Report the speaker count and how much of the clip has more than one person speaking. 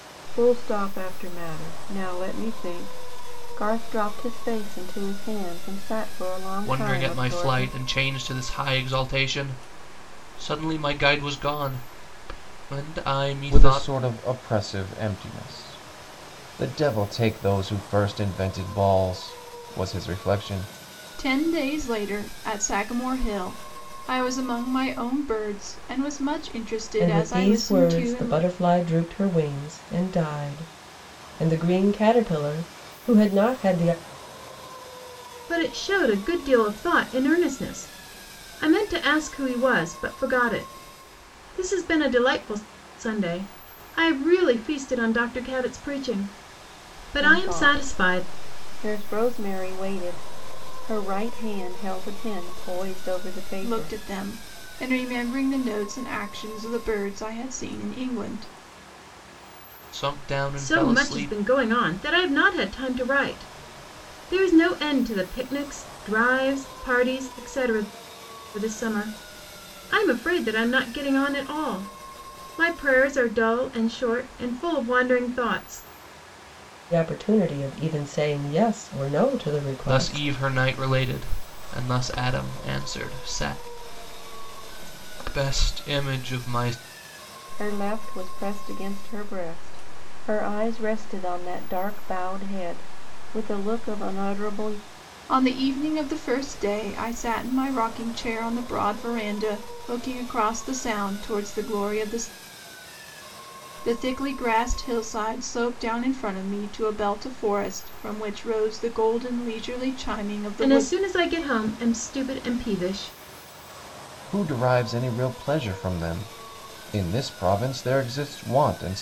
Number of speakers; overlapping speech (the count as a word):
six, about 5%